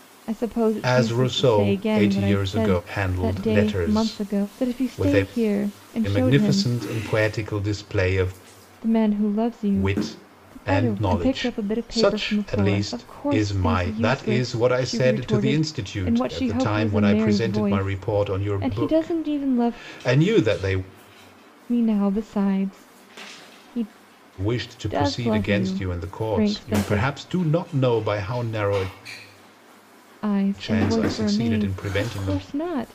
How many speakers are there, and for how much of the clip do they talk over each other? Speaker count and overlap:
2, about 58%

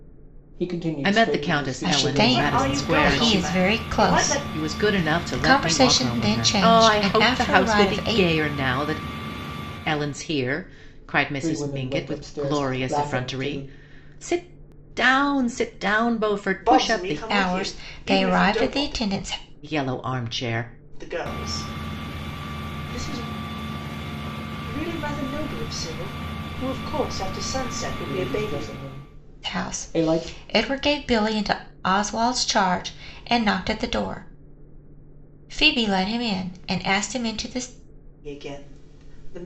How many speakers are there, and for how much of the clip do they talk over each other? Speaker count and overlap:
4, about 34%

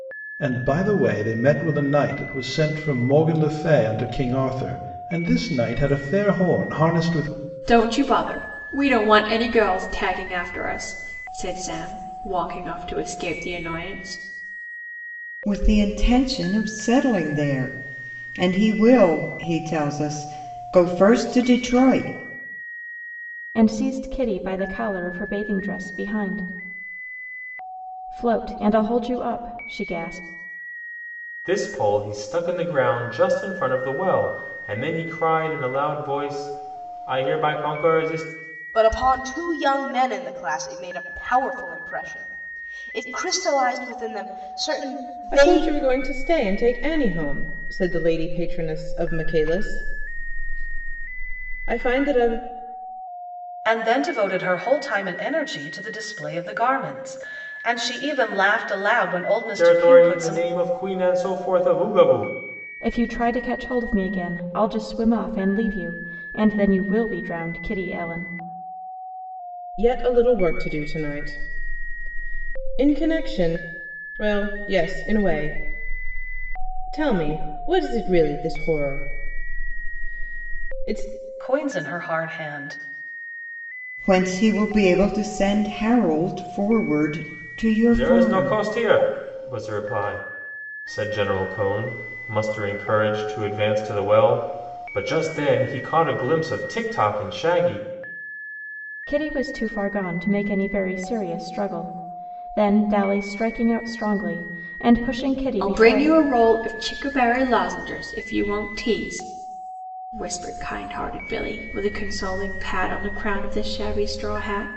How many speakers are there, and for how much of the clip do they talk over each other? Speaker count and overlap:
8, about 2%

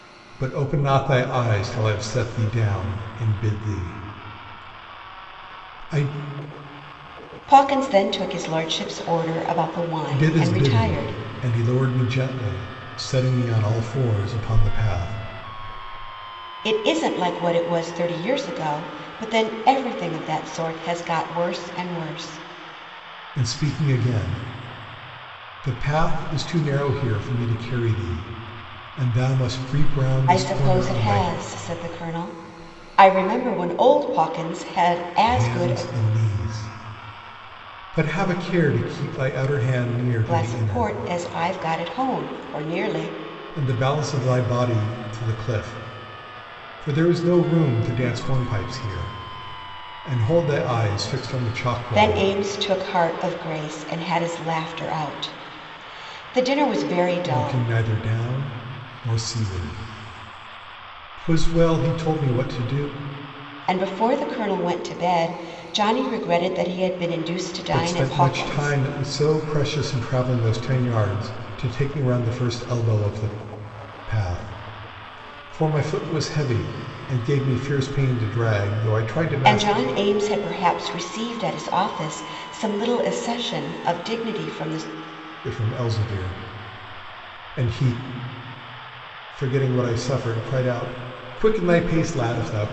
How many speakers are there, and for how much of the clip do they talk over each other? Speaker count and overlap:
2, about 6%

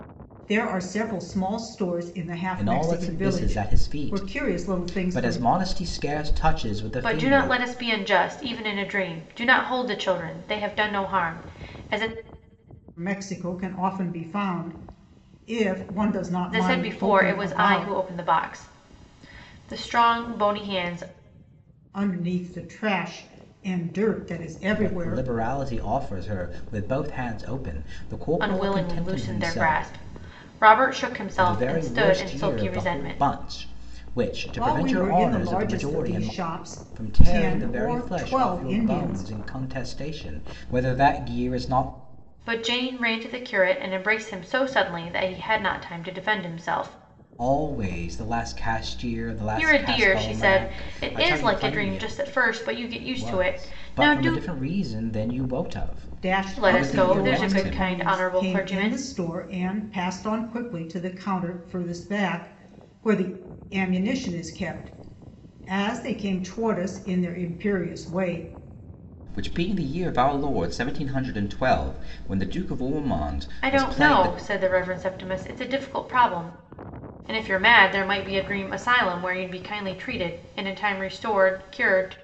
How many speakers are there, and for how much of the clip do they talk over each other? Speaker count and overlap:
3, about 25%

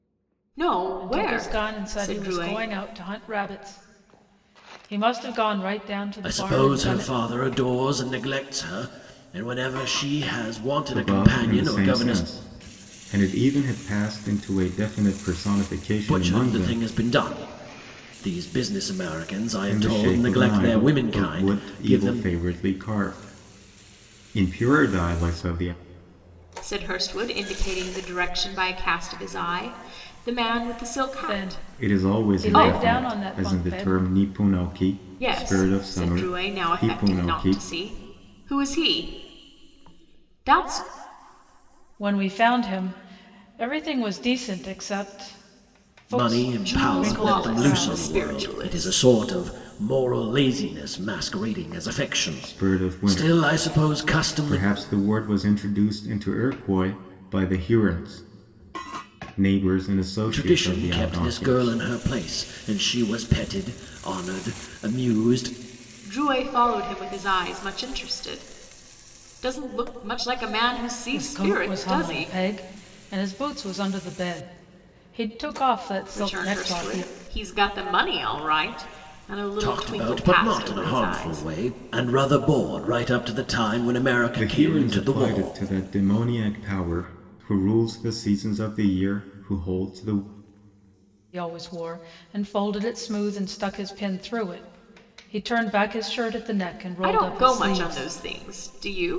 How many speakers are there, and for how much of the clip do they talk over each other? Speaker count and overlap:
4, about 26%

